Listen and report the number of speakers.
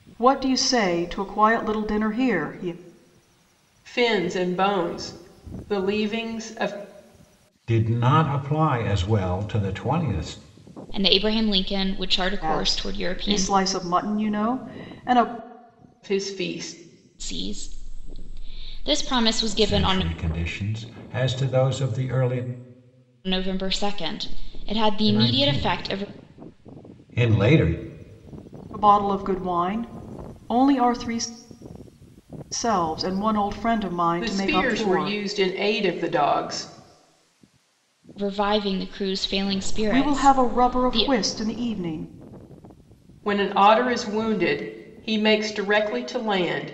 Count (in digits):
4